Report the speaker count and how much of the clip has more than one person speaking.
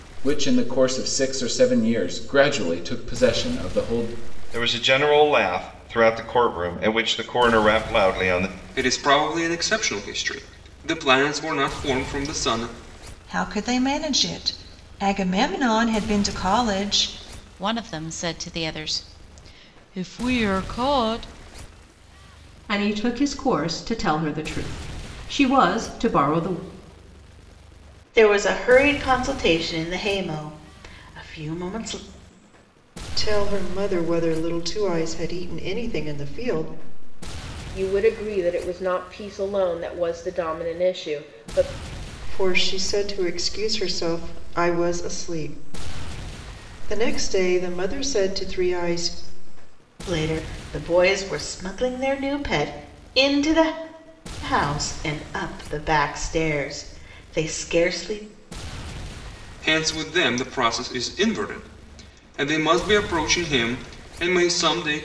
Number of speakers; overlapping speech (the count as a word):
nine, no overlap